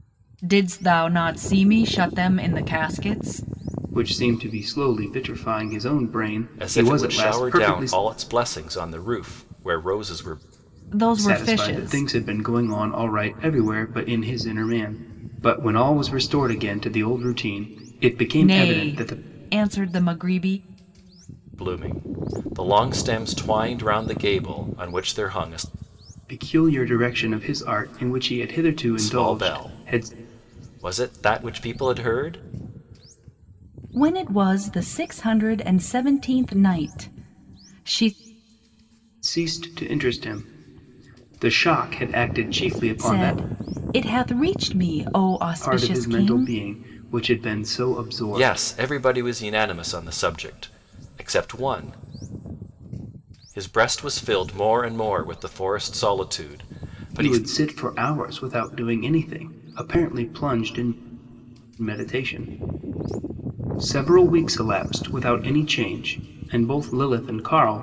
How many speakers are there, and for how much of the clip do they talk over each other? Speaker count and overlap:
three, about 9%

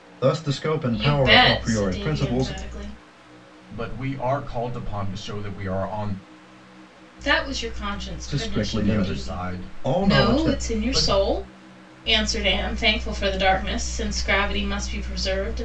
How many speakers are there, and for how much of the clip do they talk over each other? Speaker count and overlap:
three, about 29%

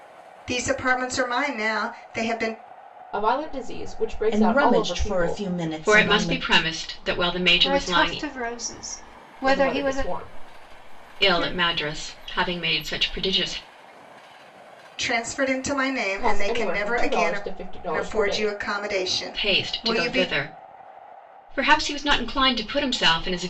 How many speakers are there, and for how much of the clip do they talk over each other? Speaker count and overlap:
five, about 27%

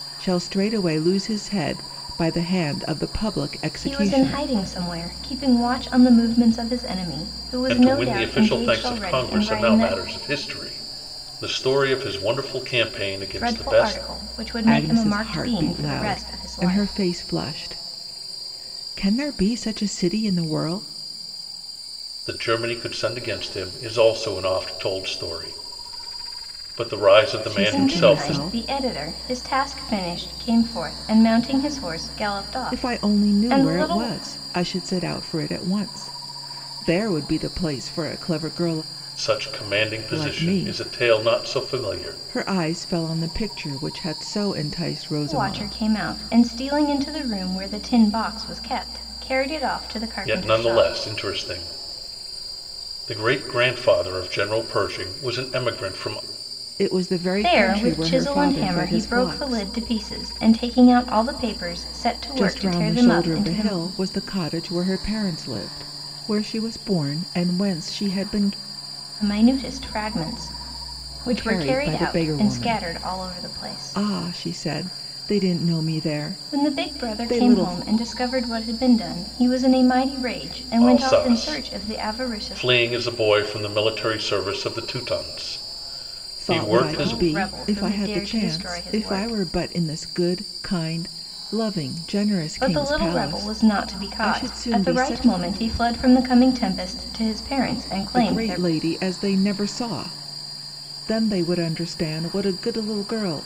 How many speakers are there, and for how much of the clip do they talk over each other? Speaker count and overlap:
three, about 28%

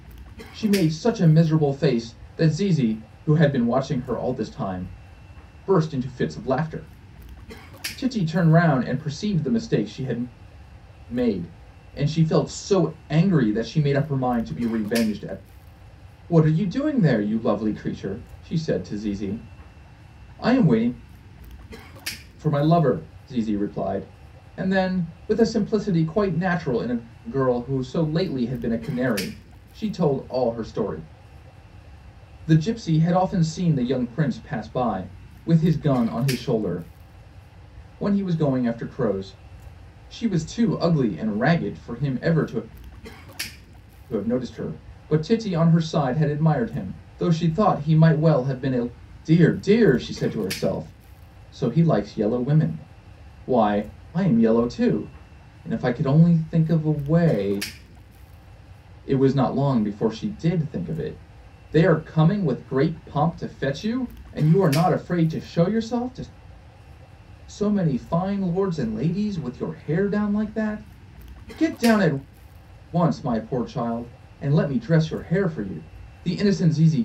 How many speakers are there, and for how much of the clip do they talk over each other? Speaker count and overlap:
one, no overlap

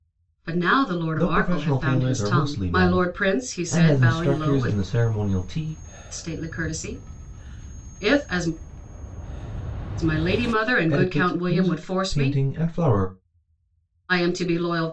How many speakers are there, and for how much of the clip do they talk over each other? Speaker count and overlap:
two, about 31%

